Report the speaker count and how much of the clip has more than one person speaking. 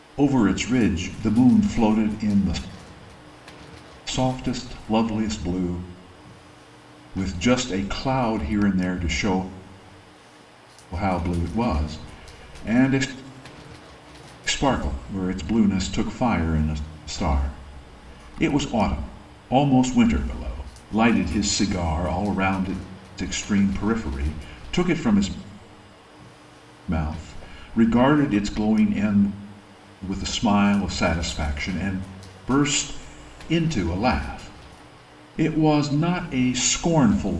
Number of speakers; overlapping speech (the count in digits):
1, no overlap